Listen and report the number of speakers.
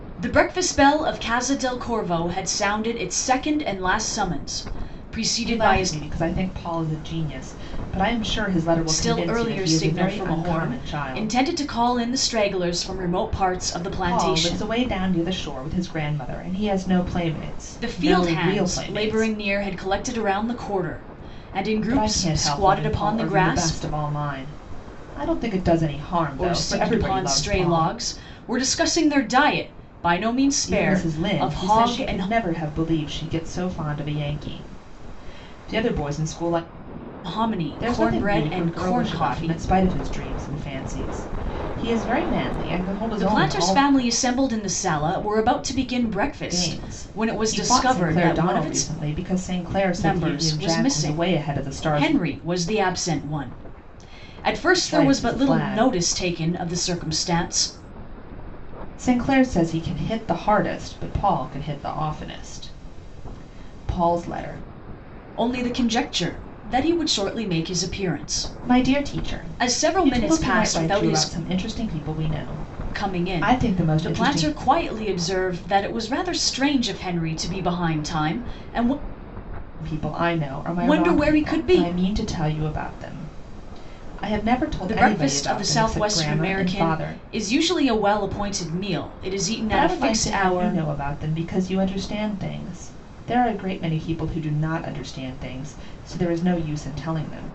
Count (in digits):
2